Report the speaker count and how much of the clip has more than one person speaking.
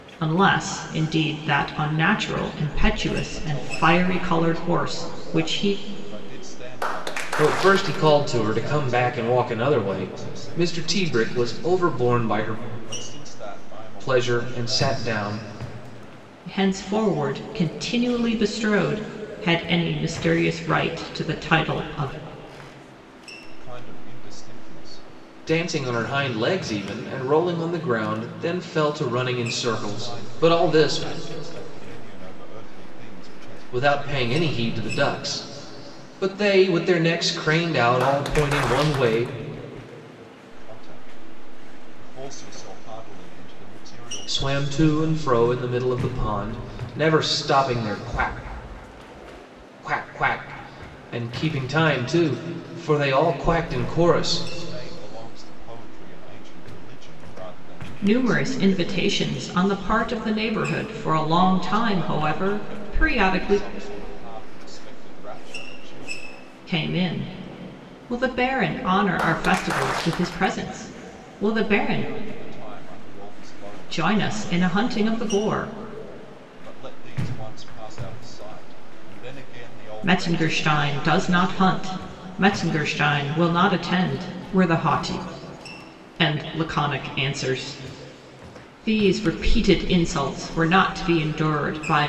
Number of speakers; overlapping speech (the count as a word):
three, about 22%